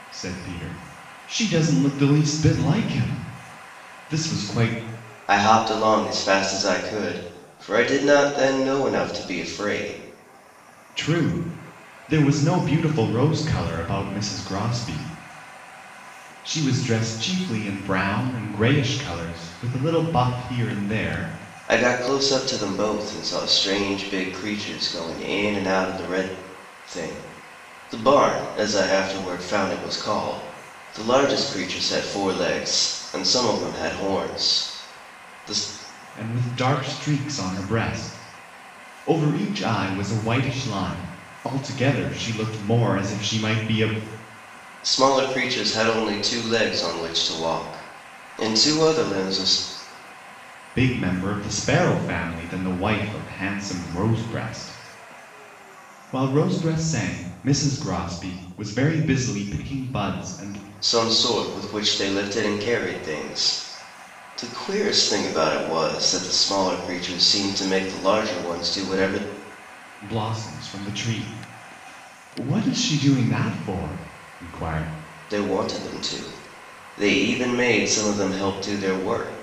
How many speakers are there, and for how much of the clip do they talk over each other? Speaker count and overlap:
2, no overlap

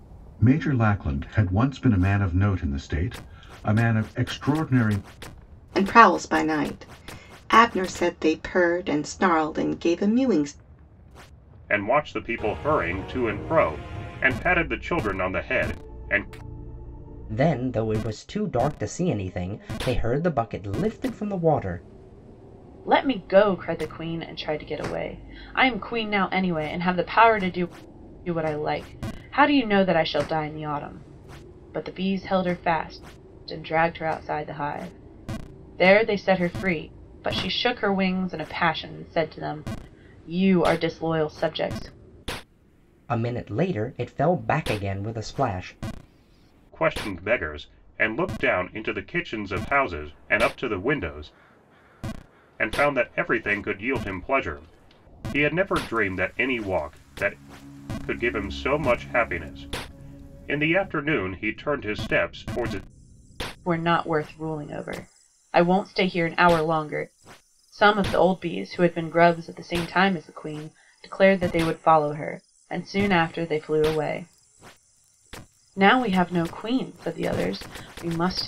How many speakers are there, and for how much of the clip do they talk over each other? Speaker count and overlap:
5, no overlap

